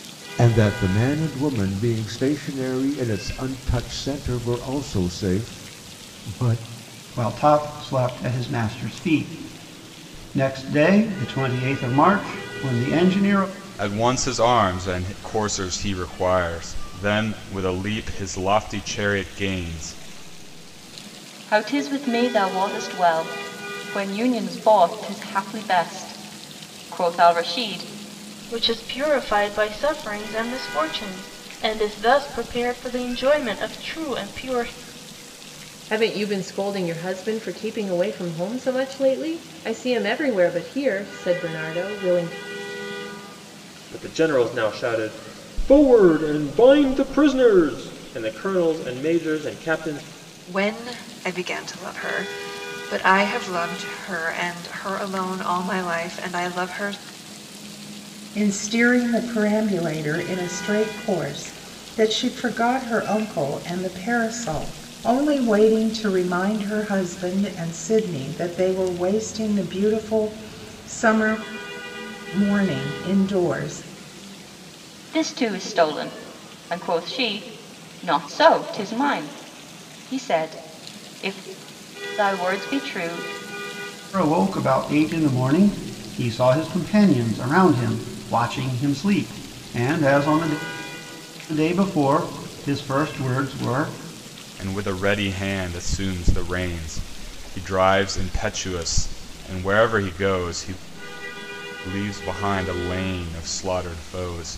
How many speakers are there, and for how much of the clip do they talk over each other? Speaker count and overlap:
9, no overlap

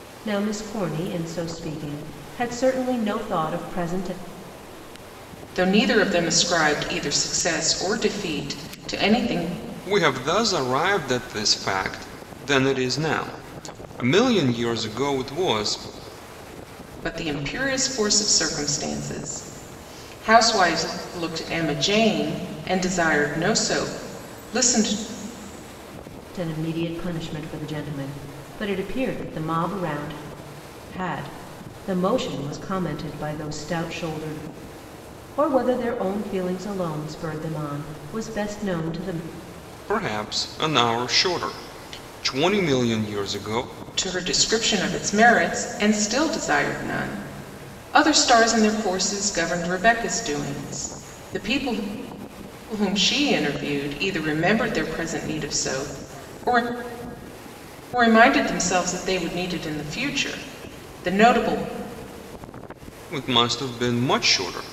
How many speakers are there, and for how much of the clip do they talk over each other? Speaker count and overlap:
3, no overlap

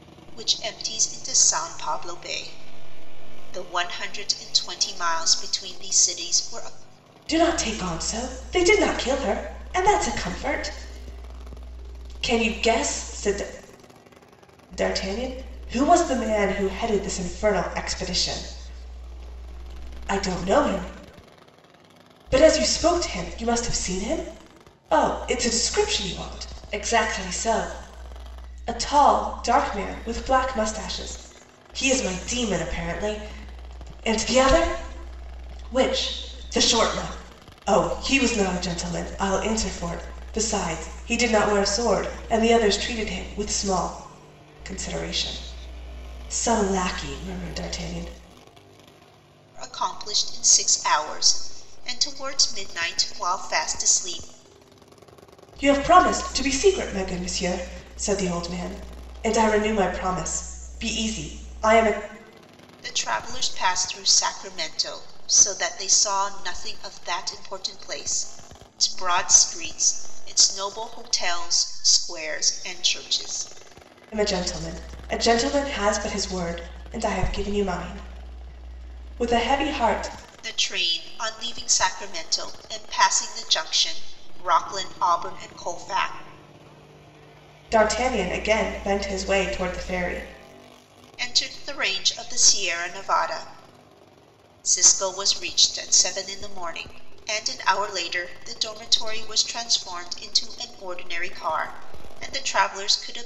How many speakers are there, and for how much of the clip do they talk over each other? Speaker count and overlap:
2, no overlap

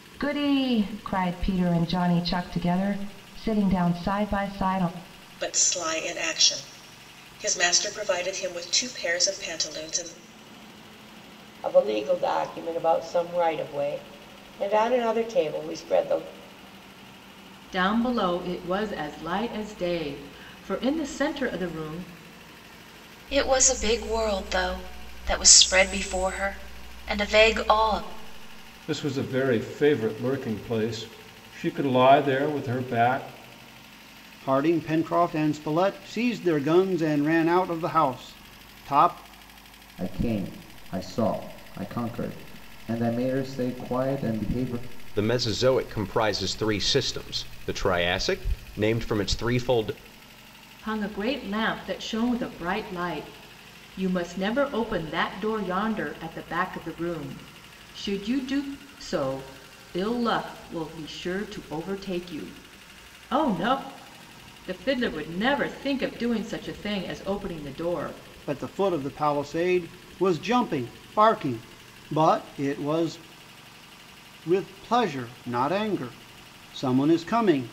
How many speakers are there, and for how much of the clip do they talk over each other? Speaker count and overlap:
9, no overlap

